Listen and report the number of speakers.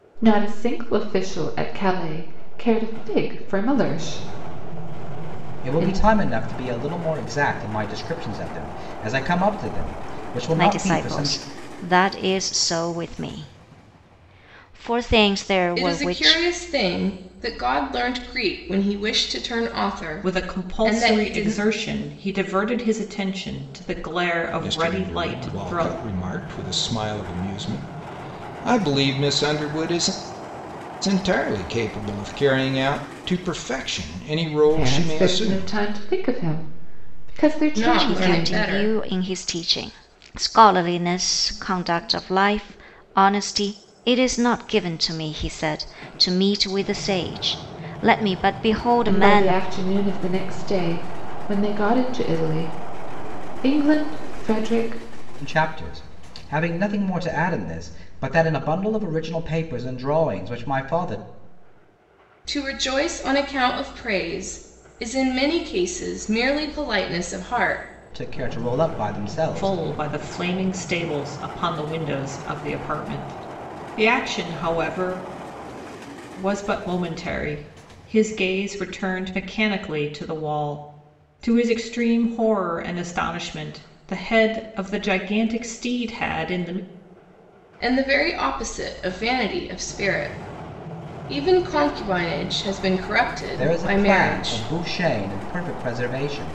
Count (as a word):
six